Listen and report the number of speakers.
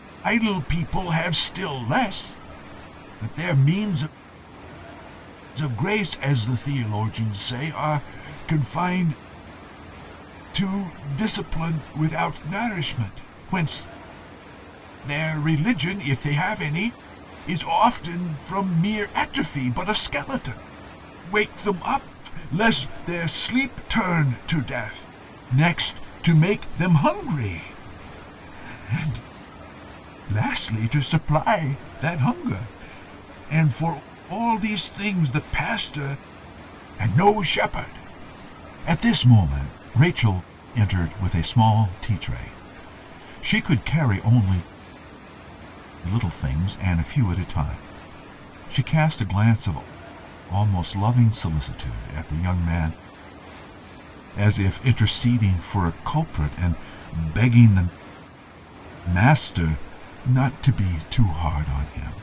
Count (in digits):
1